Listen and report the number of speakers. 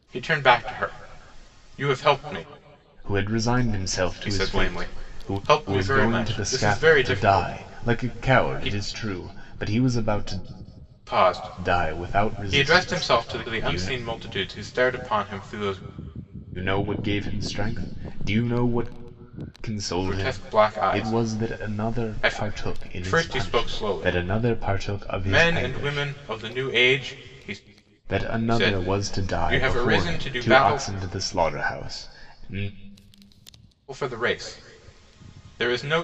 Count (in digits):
2